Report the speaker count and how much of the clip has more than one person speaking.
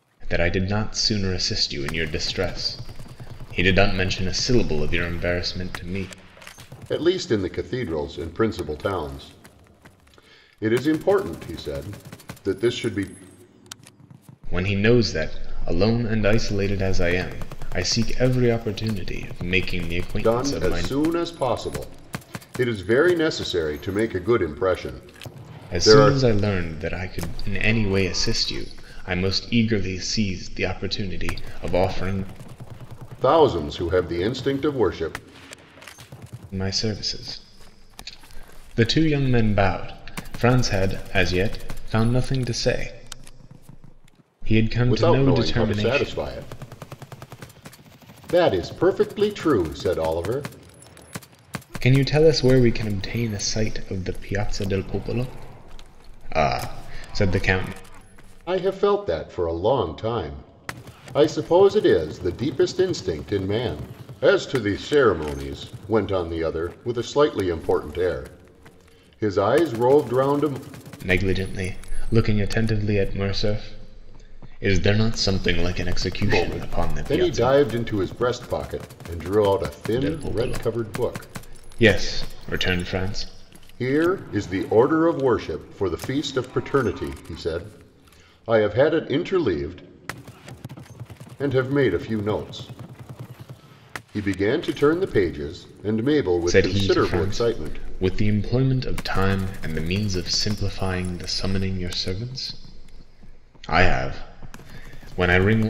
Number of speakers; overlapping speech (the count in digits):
2, about 6%